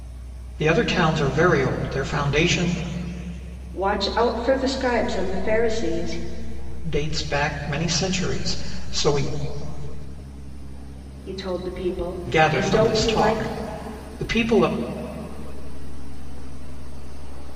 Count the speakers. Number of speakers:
3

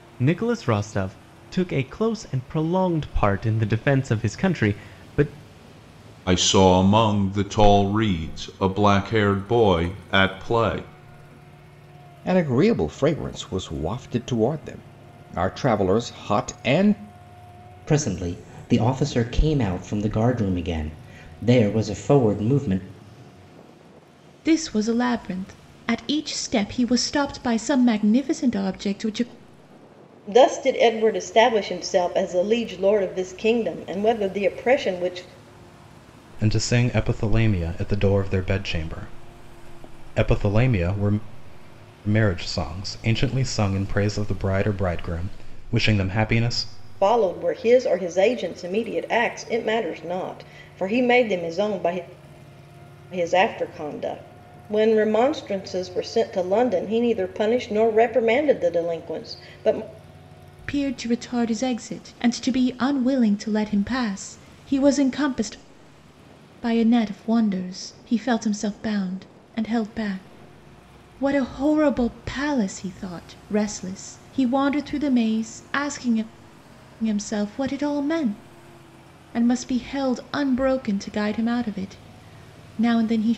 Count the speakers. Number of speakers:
7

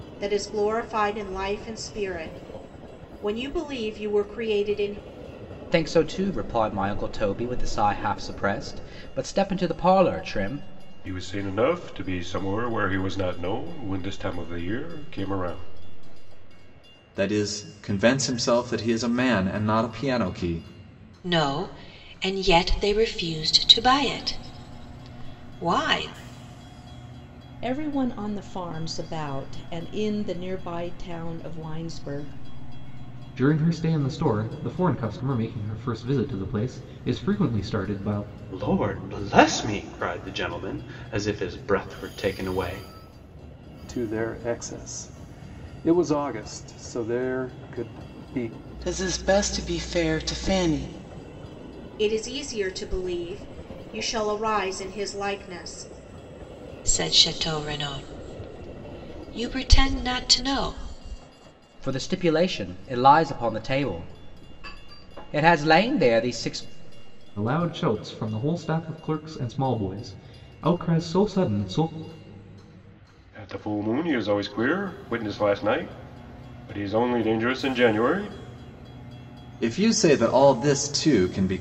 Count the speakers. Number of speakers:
10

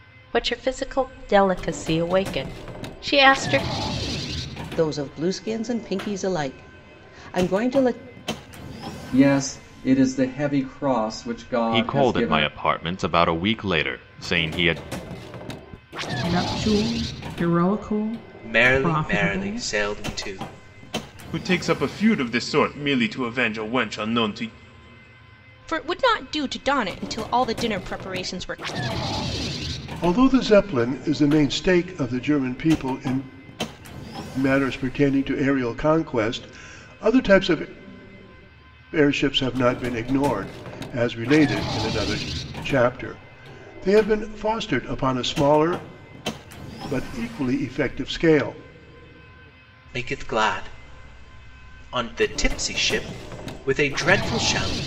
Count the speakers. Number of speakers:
9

